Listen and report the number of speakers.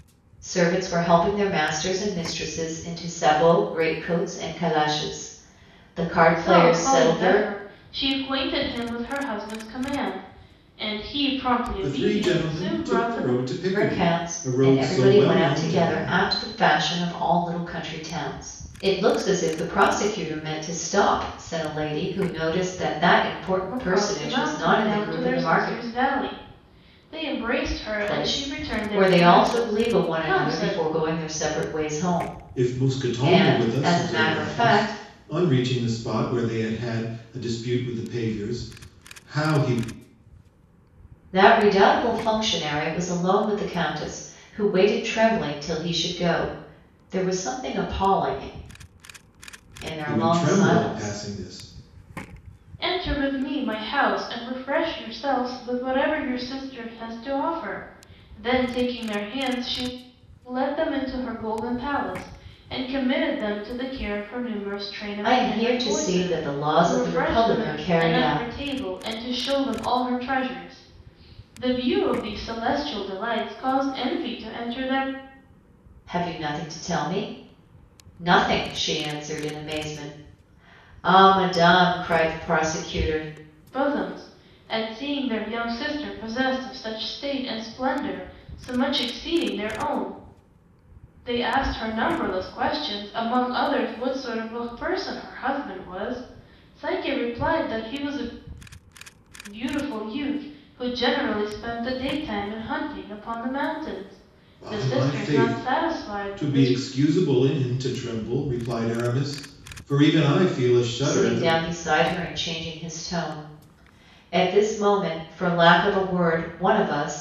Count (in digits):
3